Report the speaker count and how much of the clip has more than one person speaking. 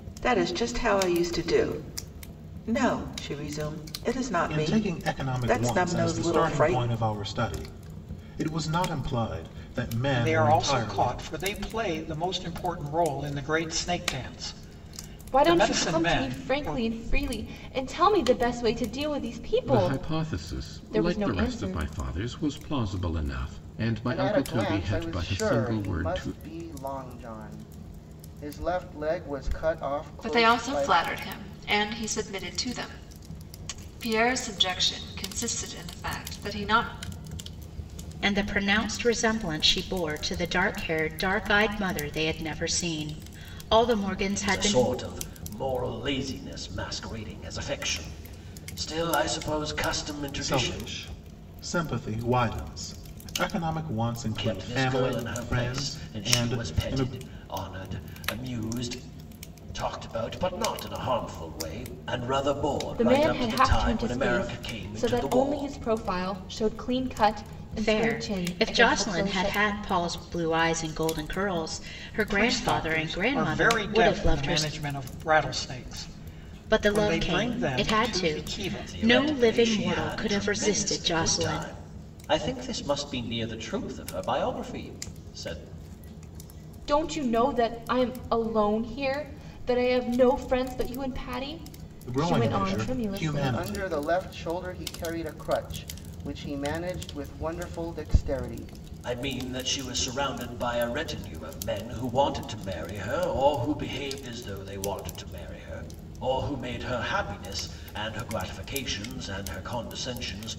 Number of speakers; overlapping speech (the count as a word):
nine, about 26%